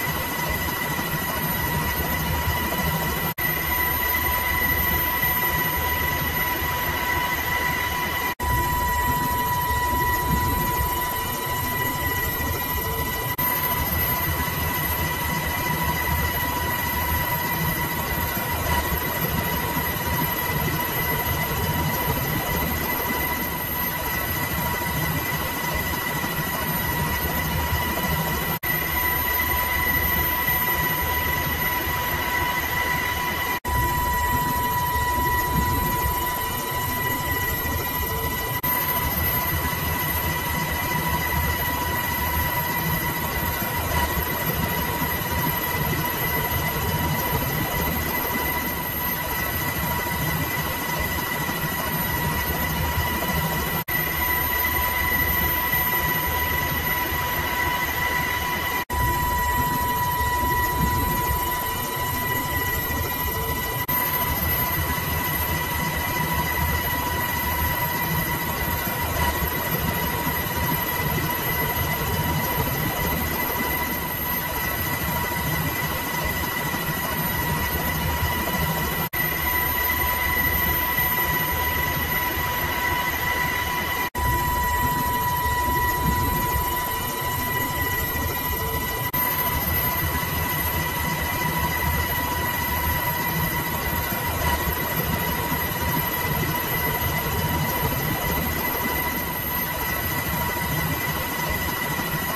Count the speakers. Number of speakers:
0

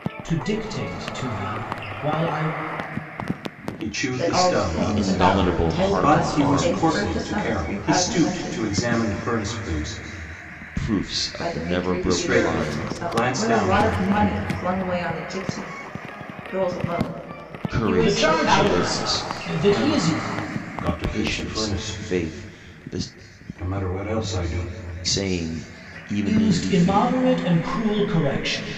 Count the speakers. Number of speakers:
4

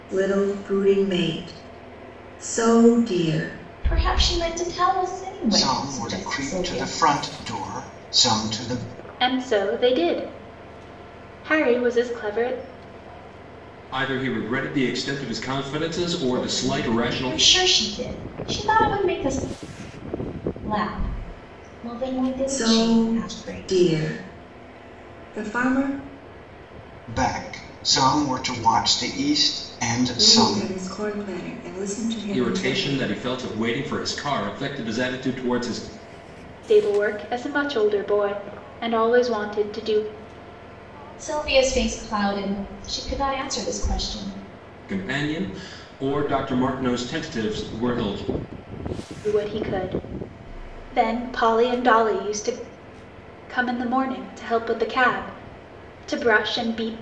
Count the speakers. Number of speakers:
5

